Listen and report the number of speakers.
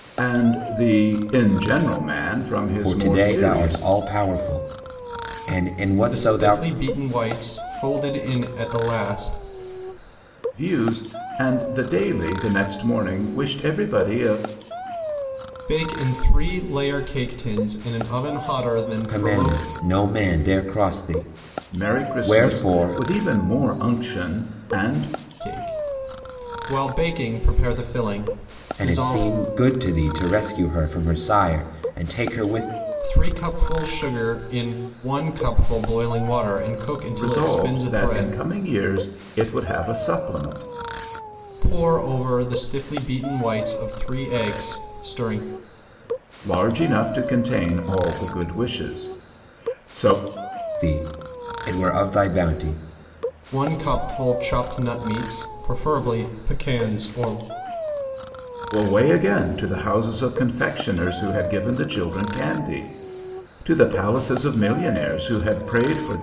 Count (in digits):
3